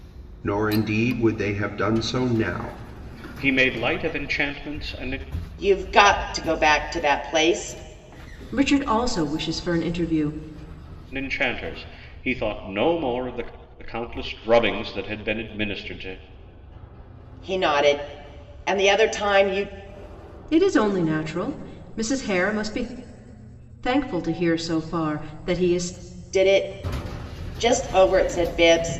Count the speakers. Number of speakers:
four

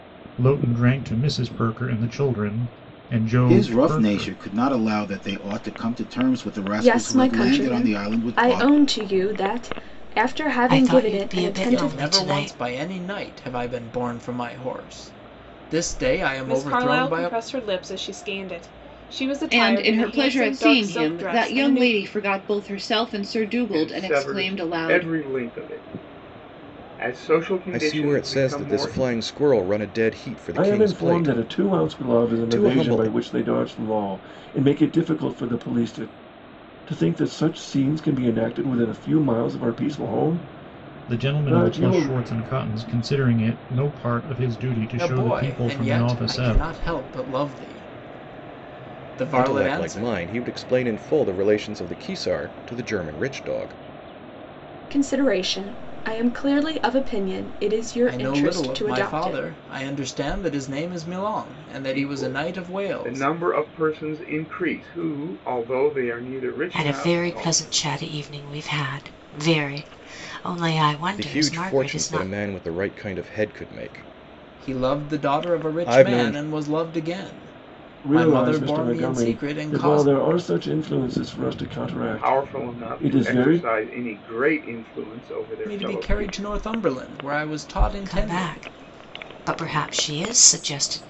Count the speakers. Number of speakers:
ten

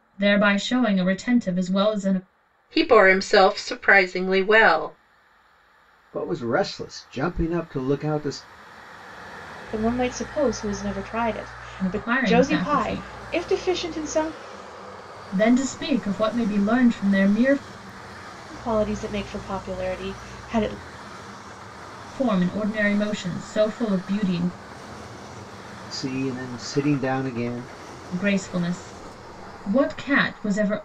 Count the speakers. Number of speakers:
four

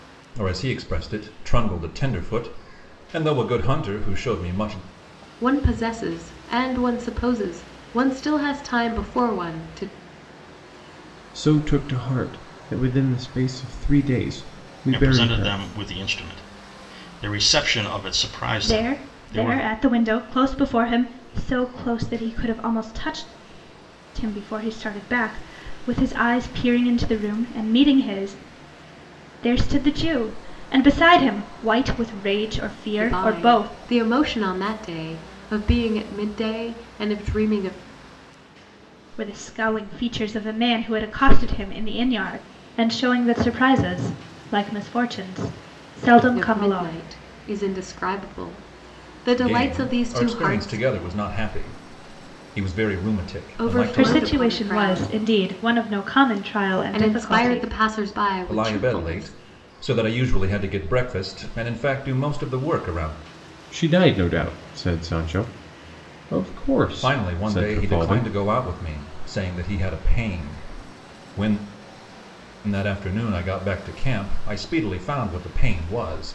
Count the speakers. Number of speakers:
five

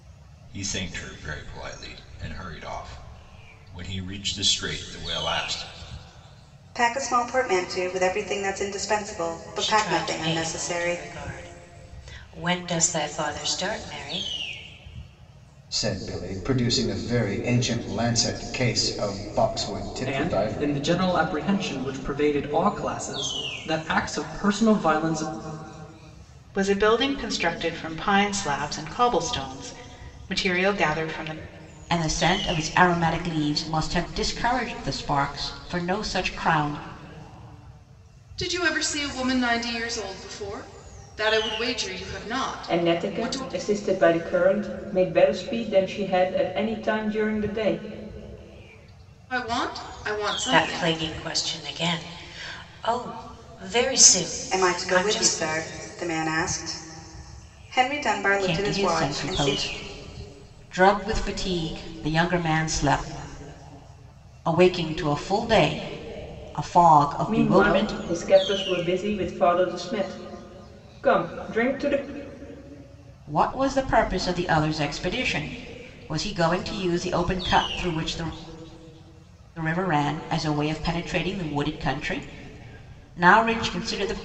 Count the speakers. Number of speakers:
nine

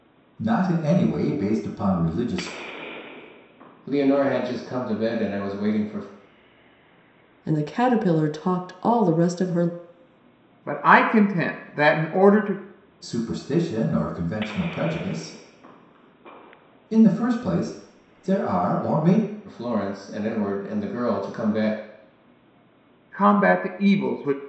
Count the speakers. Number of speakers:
four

